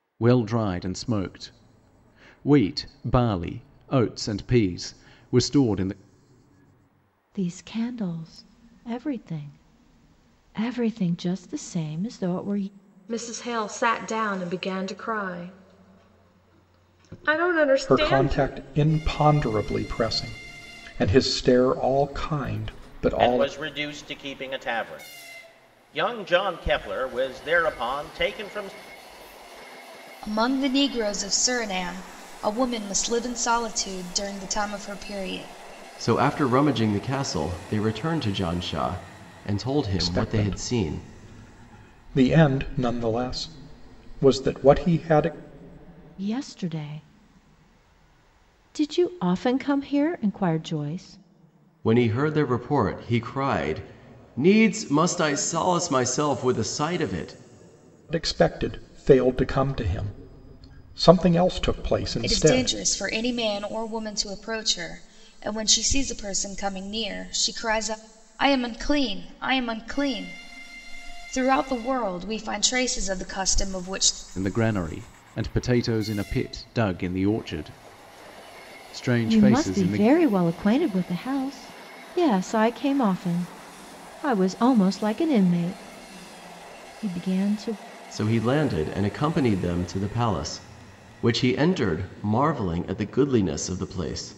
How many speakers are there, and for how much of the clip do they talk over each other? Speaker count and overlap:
7, about 4%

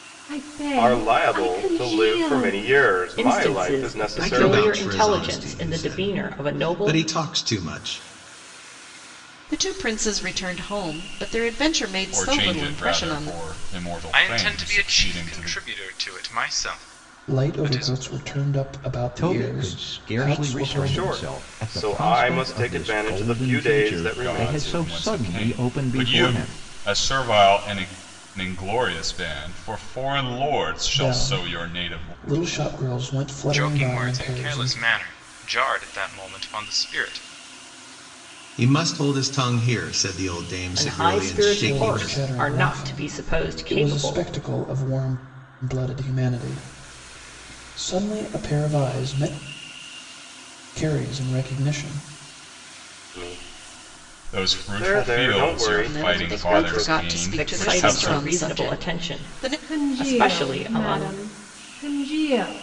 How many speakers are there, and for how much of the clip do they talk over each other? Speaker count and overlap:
9, about 48%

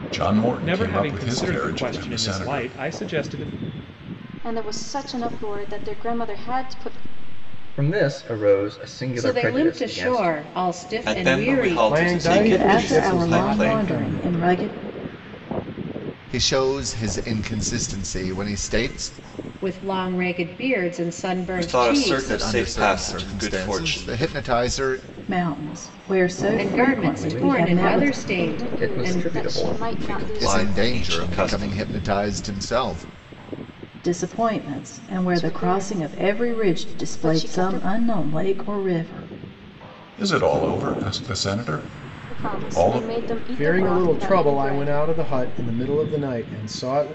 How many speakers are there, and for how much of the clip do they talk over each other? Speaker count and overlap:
9, about 41%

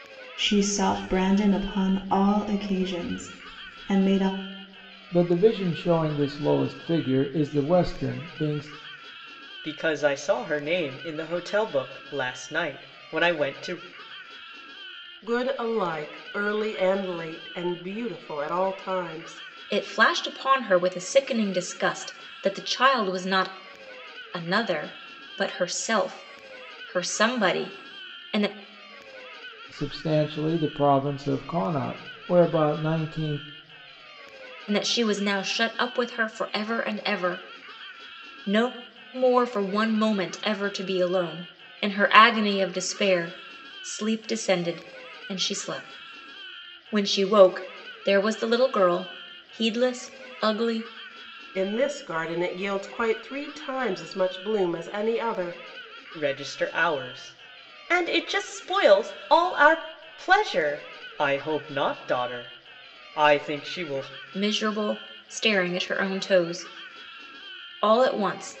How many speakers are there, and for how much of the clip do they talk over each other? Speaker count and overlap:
5, no overlap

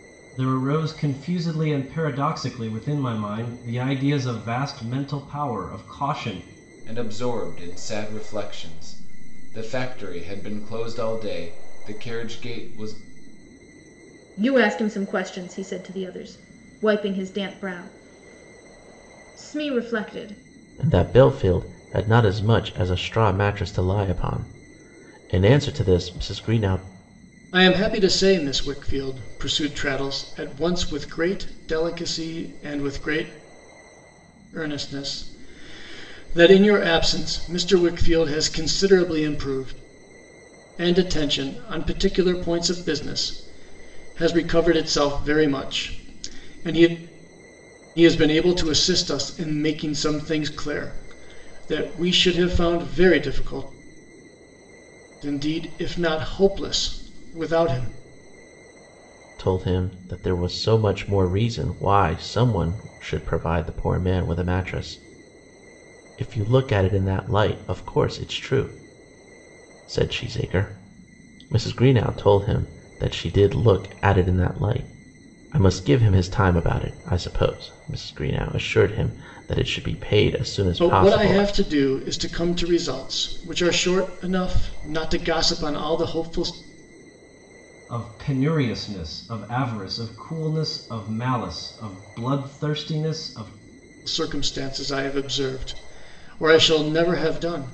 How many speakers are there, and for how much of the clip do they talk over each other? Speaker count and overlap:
5, about 1%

